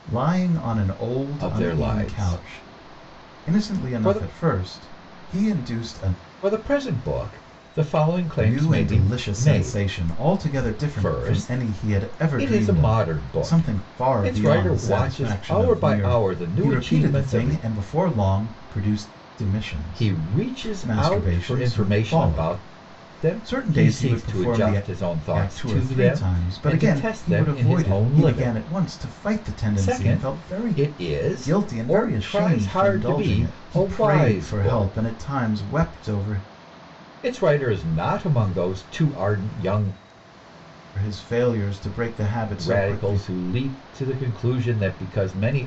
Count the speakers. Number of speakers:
2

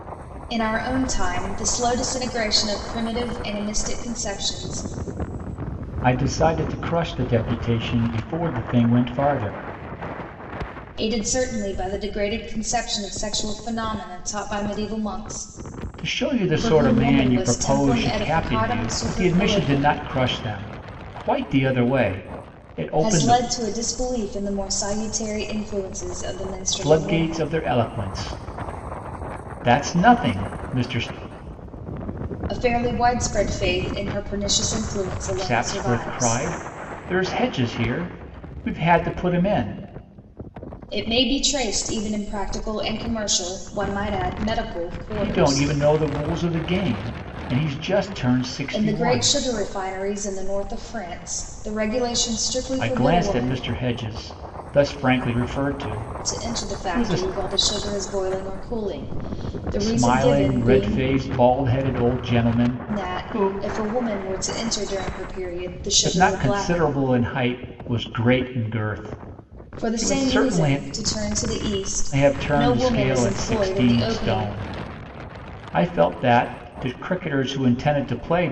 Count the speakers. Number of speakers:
2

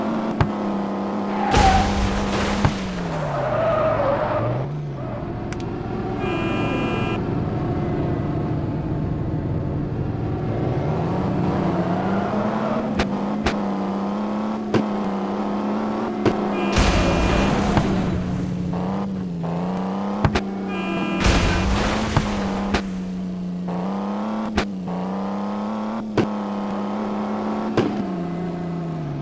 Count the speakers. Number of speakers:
0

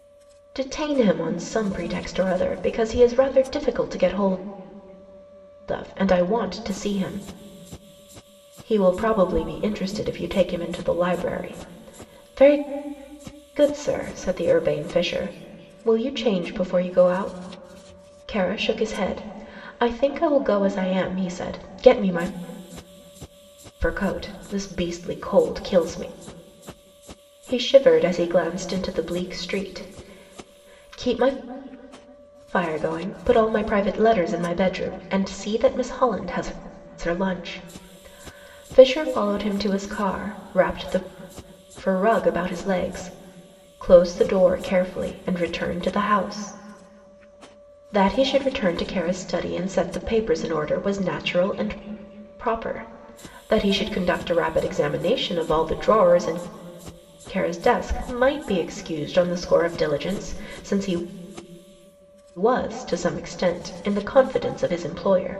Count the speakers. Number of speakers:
1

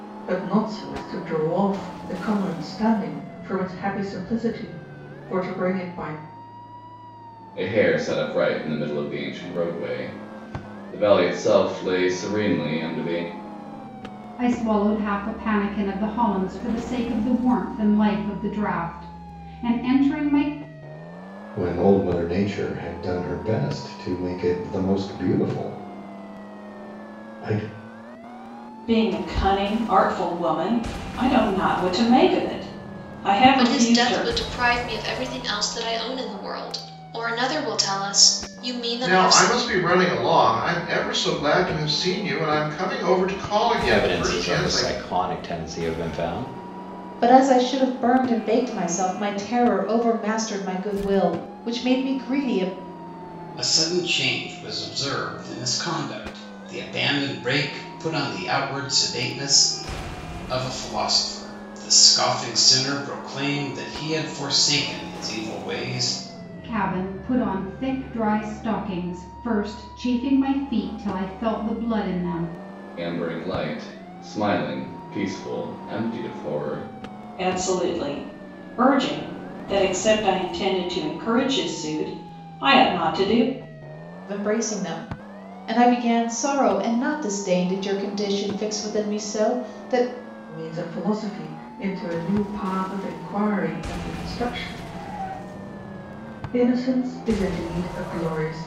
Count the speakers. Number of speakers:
10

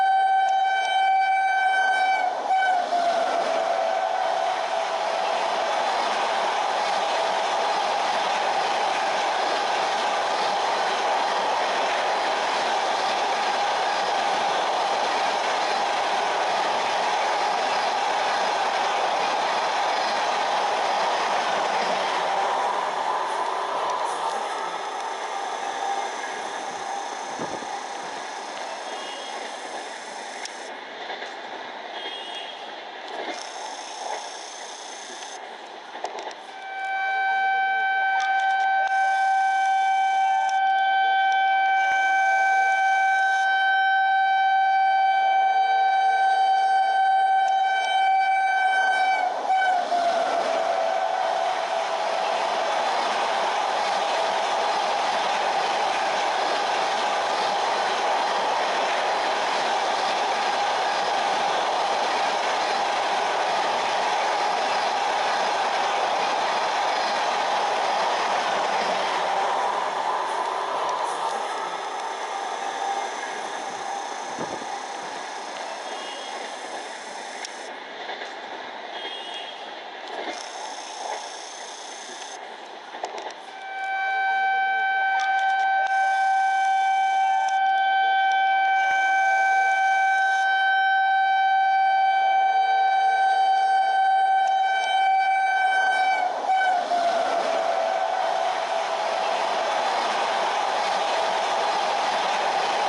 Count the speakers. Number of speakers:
0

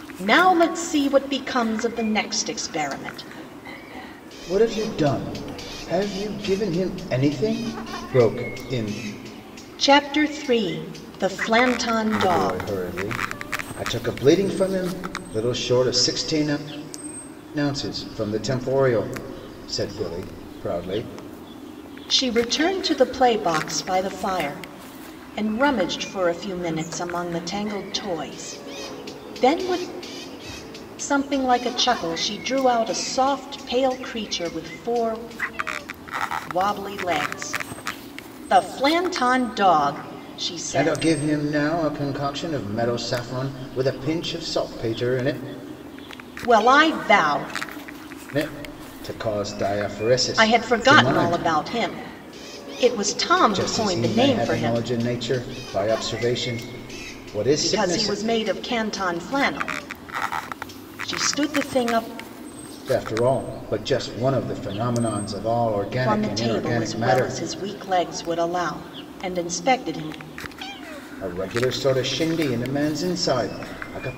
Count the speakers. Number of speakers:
2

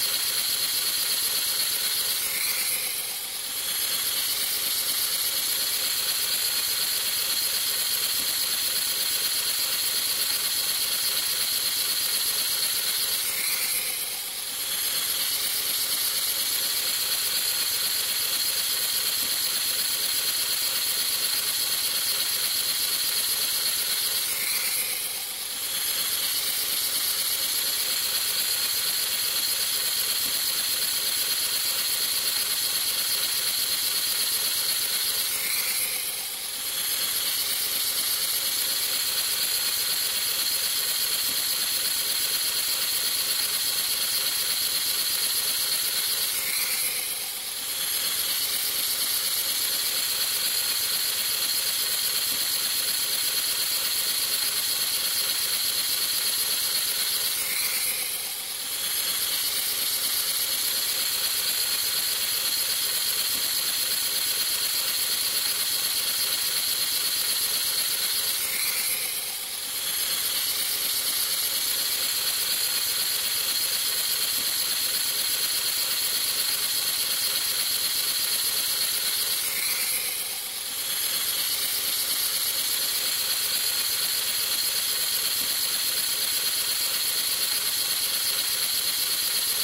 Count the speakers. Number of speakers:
0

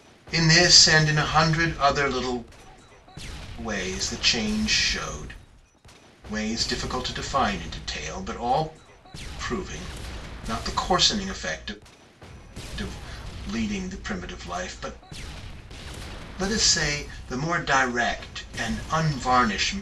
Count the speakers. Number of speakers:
1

